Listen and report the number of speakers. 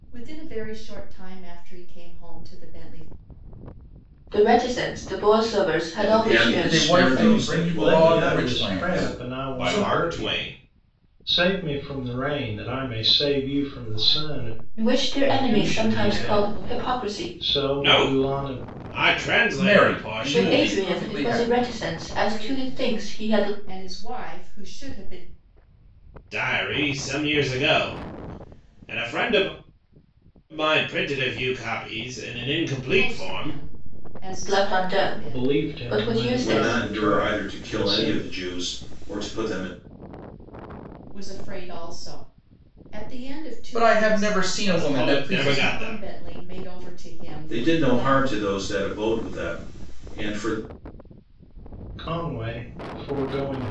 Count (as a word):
six